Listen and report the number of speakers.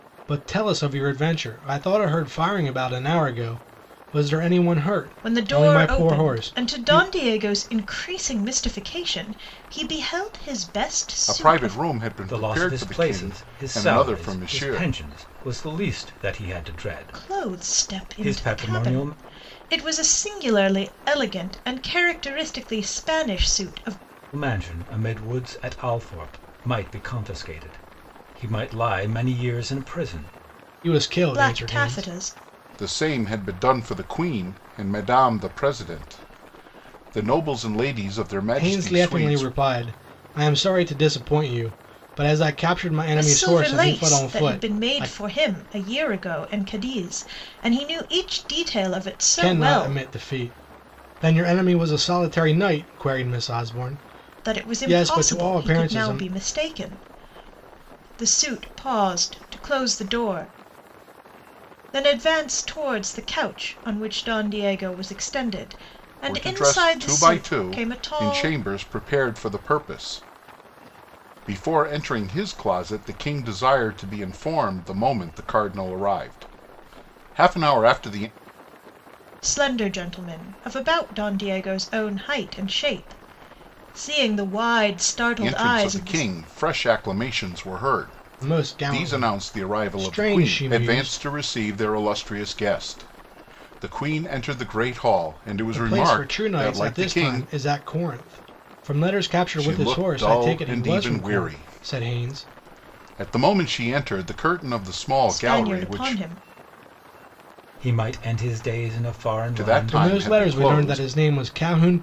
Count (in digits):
4